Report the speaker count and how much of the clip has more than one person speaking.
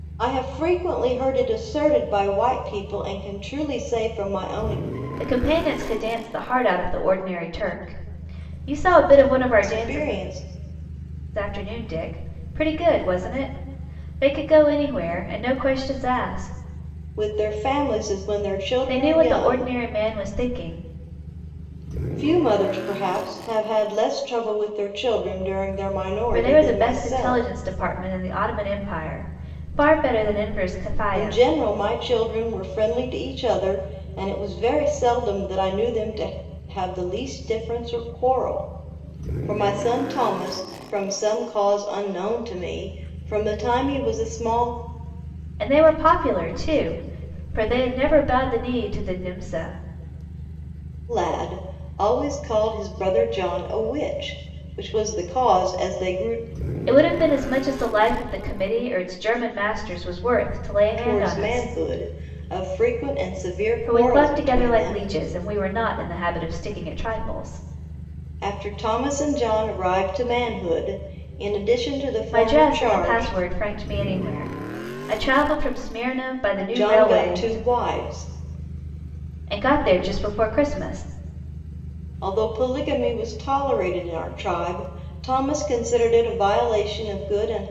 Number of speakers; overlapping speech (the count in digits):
2, about 8%